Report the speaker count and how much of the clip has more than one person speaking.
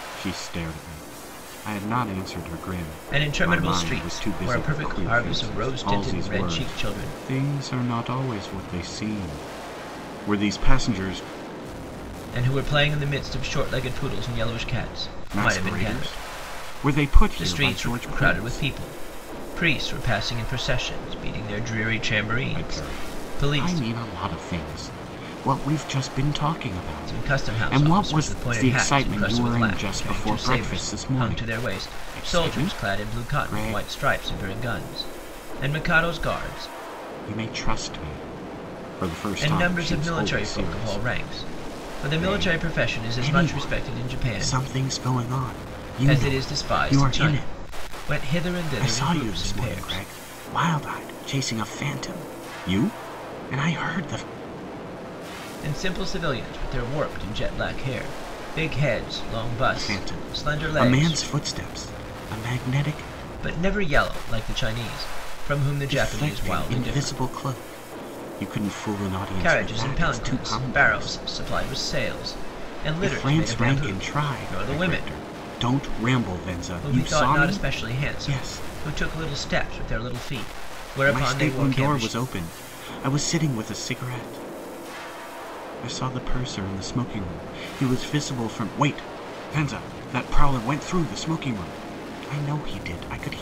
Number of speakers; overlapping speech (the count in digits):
2, about 34%